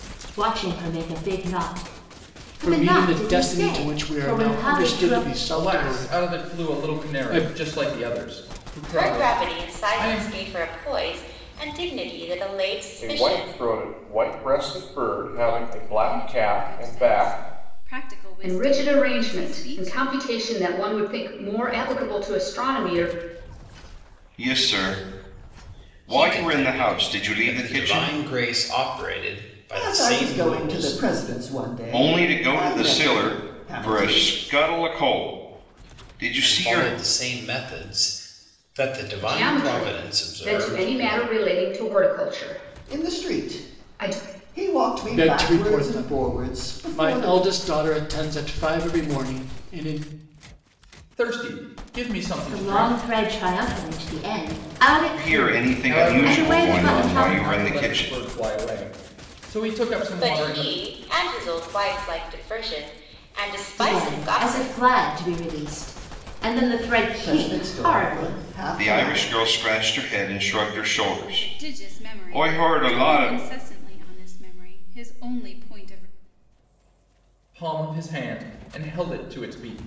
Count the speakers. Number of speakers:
10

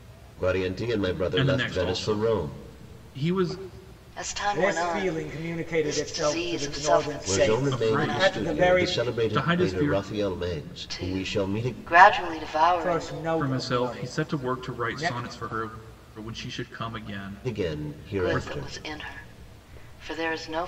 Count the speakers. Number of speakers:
4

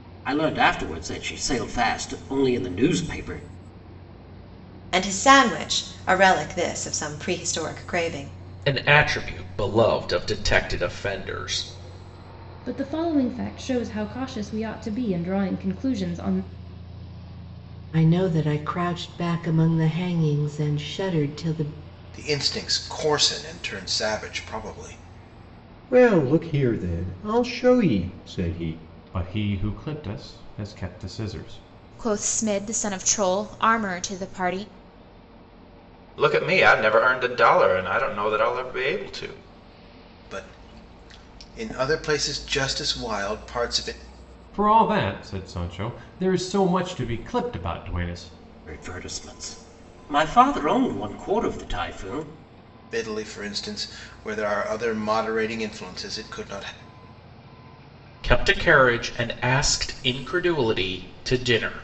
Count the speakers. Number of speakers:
10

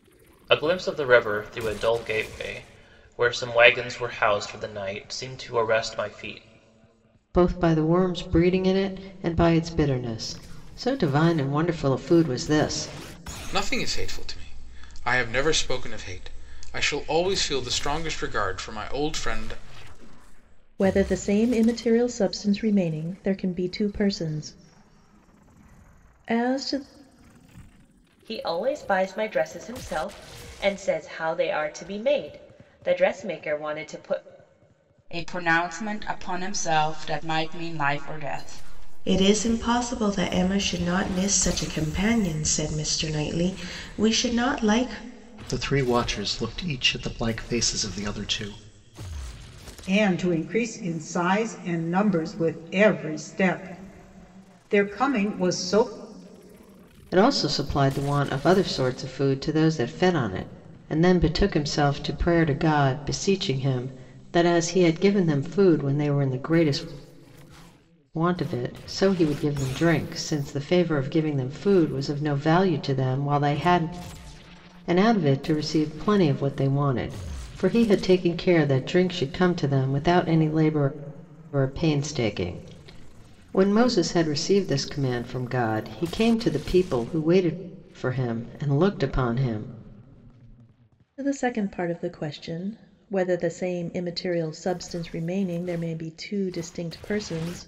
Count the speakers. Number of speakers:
9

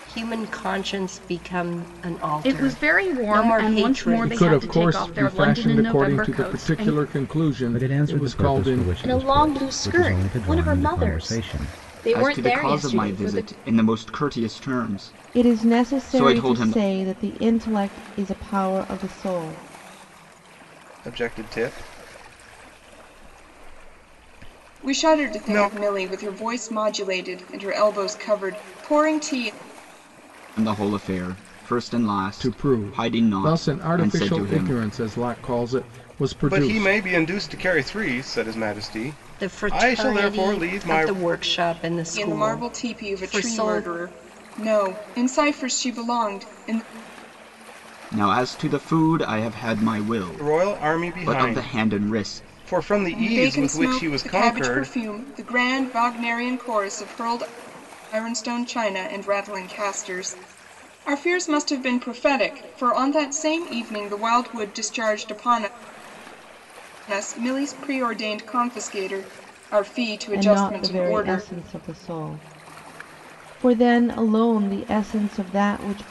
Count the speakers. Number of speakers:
9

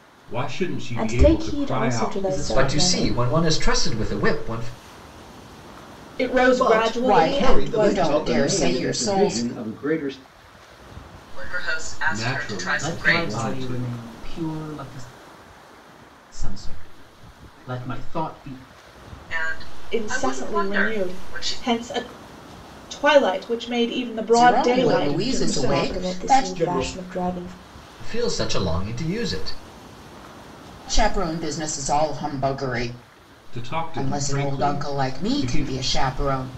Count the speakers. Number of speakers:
9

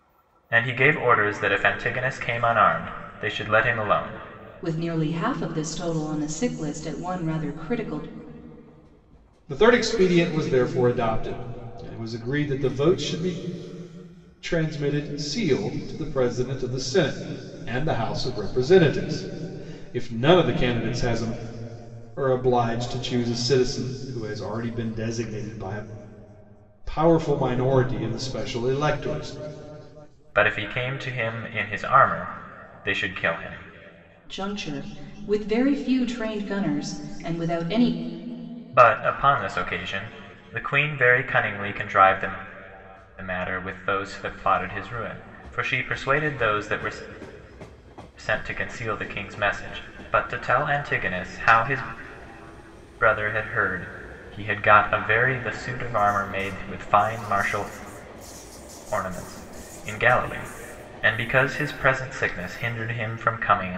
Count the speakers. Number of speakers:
3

